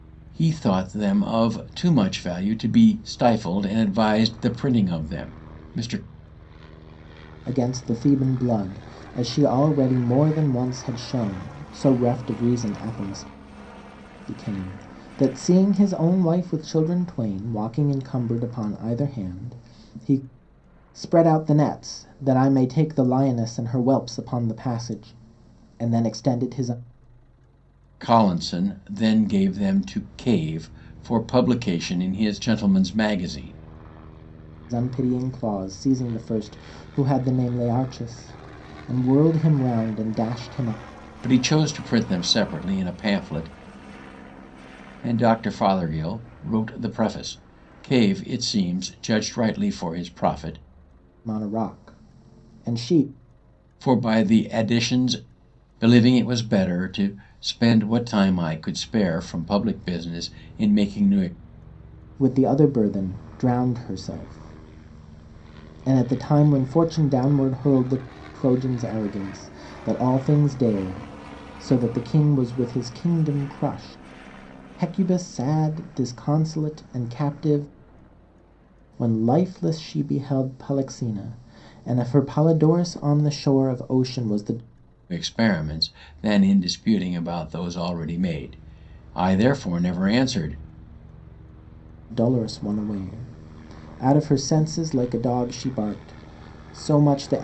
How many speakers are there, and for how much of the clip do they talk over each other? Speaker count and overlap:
two, no overlap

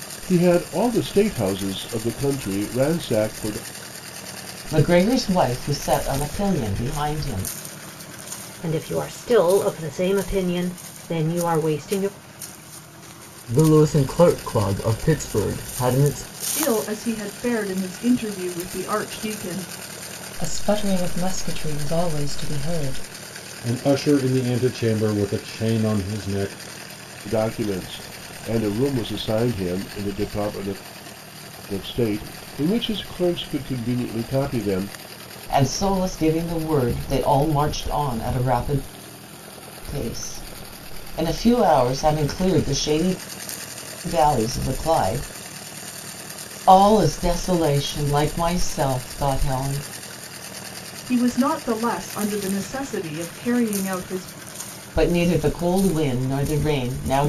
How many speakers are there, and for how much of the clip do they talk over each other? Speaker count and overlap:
seven, no overlap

